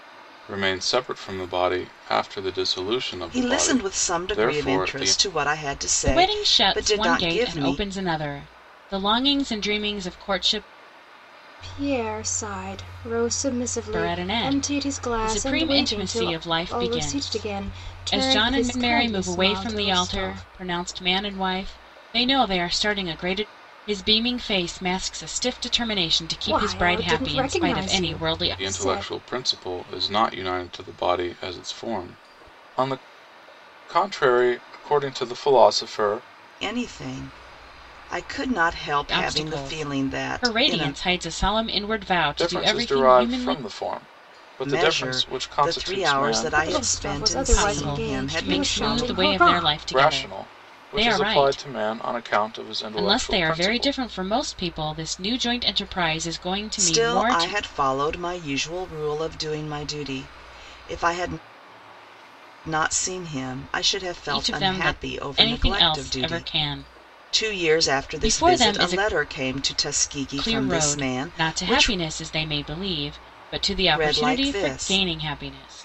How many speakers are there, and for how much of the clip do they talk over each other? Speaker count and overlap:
4, about 41%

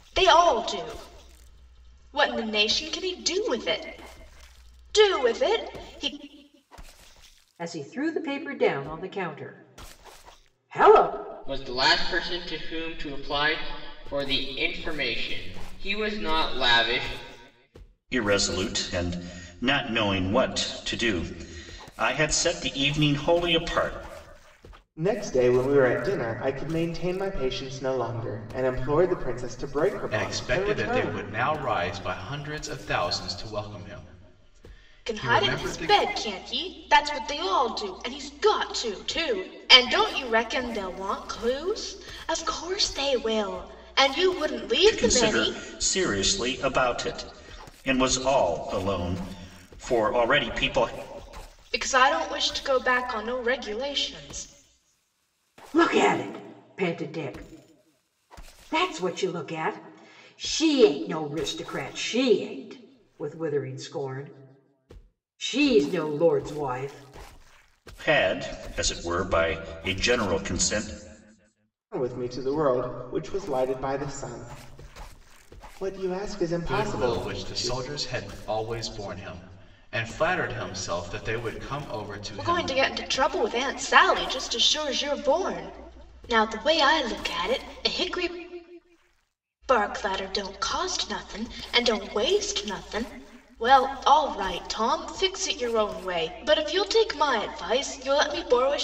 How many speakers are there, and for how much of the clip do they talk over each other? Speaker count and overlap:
6, about 4%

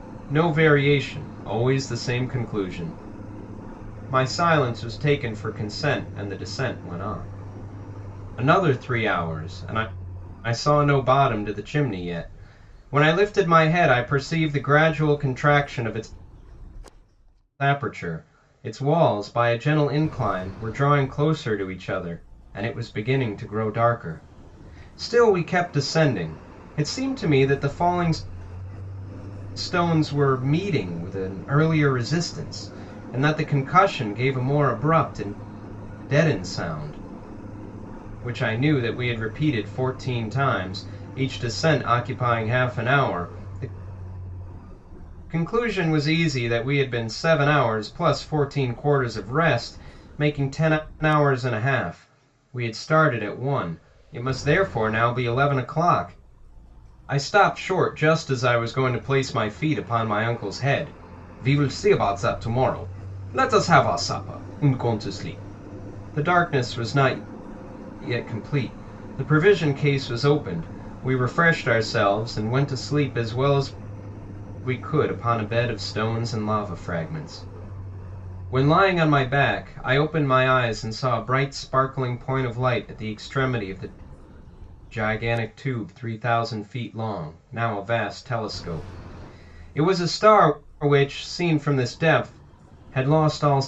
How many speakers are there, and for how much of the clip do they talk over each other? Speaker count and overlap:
1, no overlap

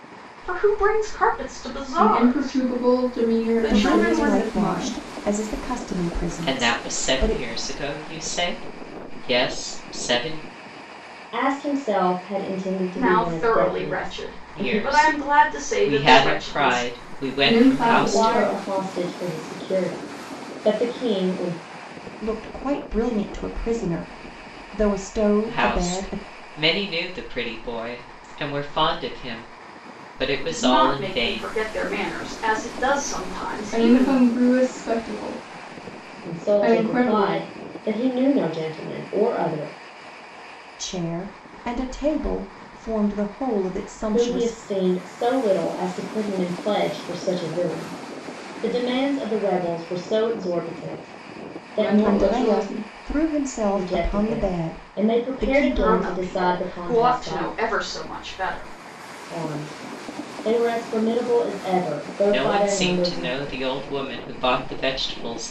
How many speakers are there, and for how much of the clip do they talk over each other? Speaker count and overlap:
5, about 30%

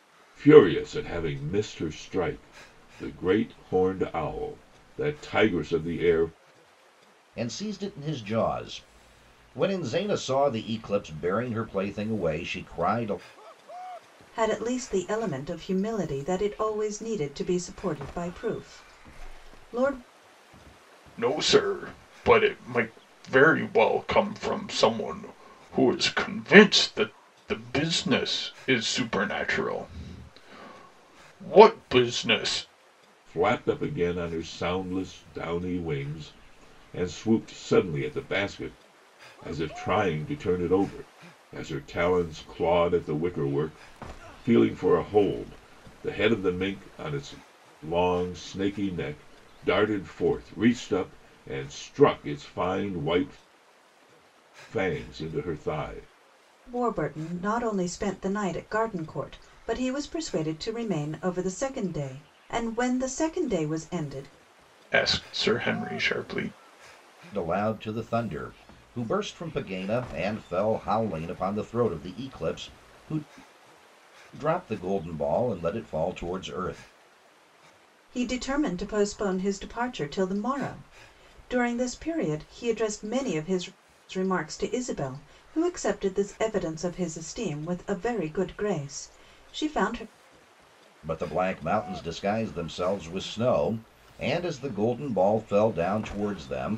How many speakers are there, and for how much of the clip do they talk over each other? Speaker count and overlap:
4, no overlap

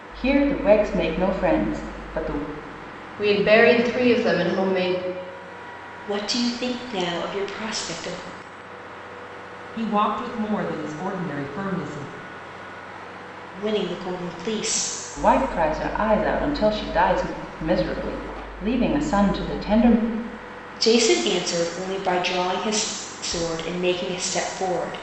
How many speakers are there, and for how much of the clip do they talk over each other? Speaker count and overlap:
4, no overlap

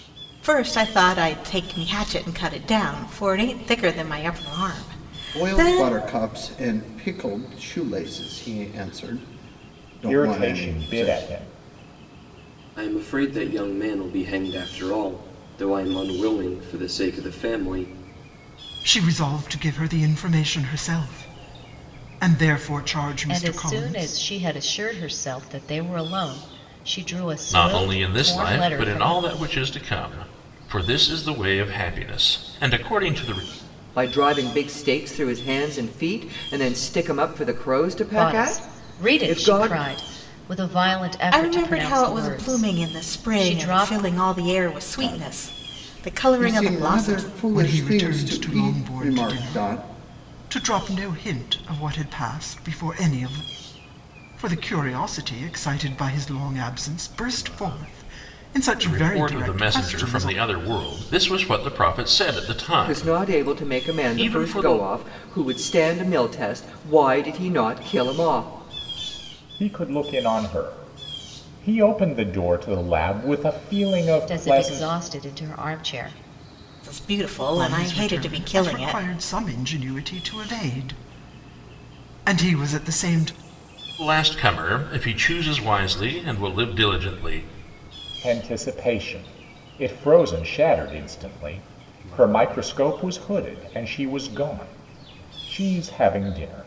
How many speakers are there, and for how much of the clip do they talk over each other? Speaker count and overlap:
8, about 20%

